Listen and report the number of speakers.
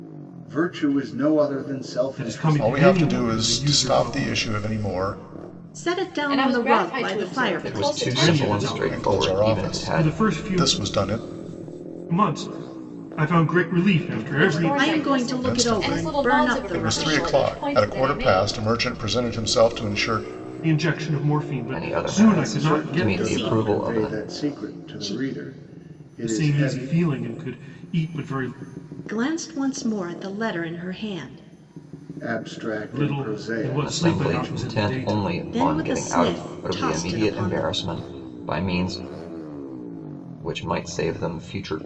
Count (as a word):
six